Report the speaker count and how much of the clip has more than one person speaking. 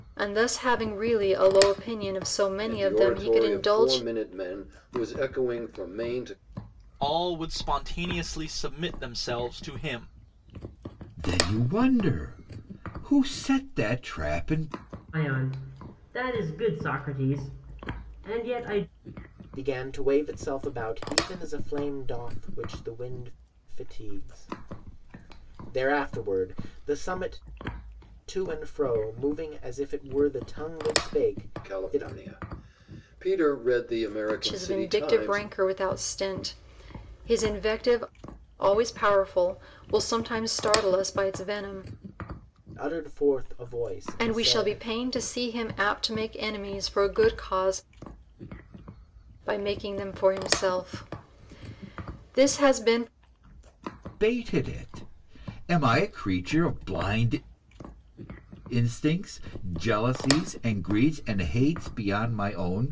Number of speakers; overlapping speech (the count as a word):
six, about 6%